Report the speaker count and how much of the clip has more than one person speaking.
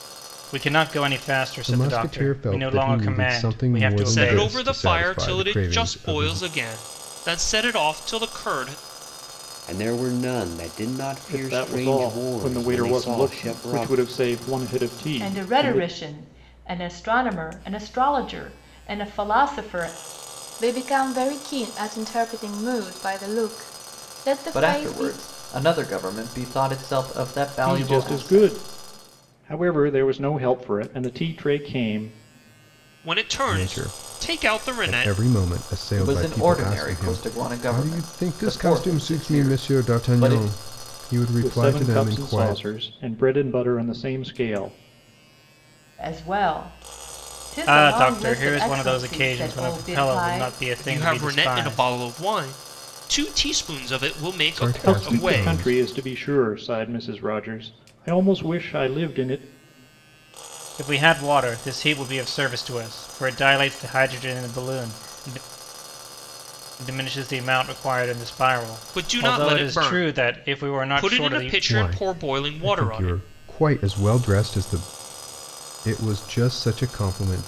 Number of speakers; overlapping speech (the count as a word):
eight, about 35%